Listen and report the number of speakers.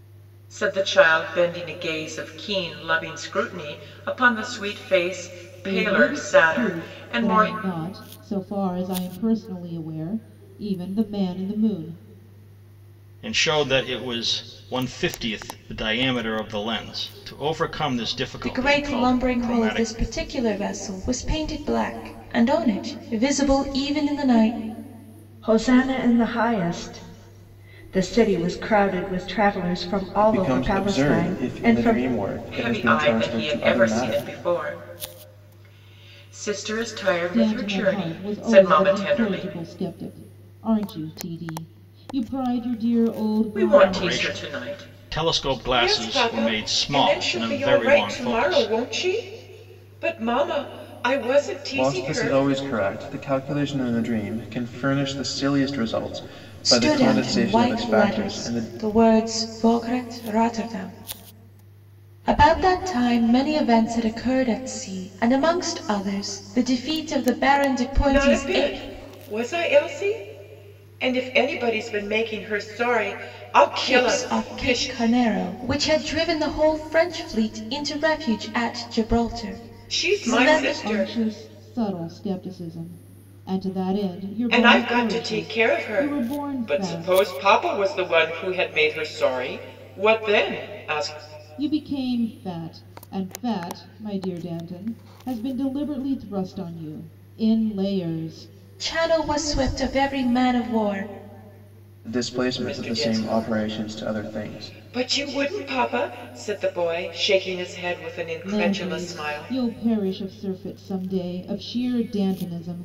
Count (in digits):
6